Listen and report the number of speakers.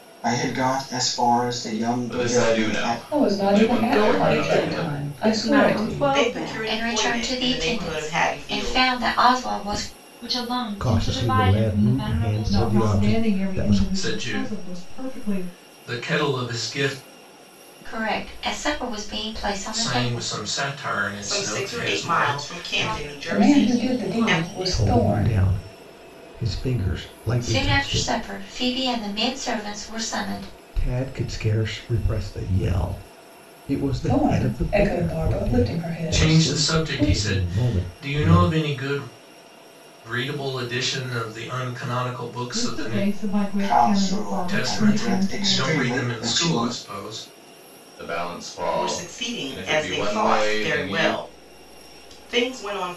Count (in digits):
10